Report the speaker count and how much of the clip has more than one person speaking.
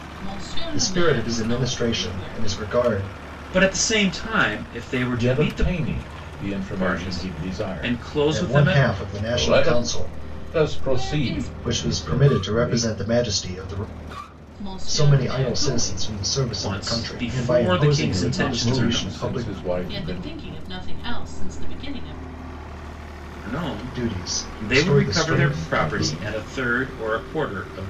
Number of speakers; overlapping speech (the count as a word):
four, about 56%